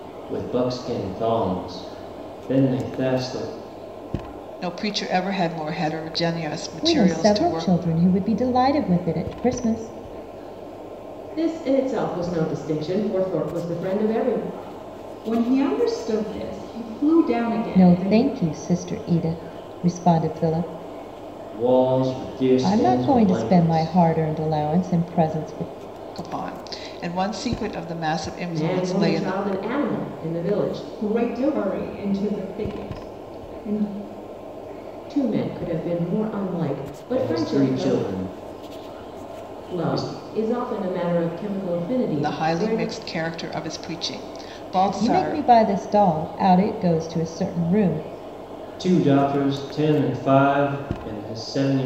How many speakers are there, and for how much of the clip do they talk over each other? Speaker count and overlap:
five, about 14%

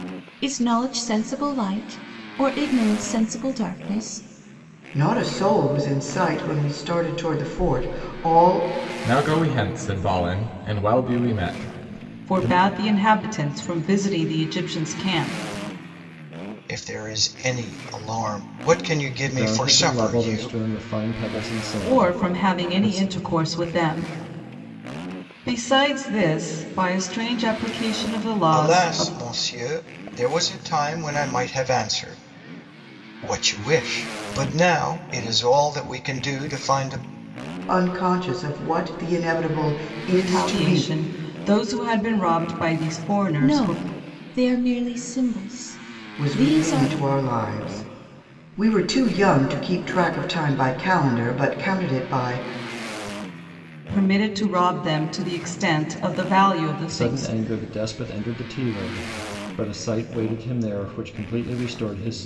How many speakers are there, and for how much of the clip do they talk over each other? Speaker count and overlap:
six, about 10%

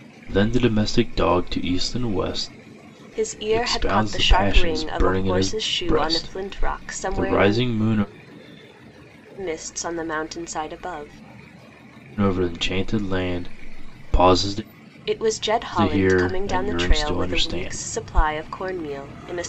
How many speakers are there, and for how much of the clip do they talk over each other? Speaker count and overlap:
two, about 31%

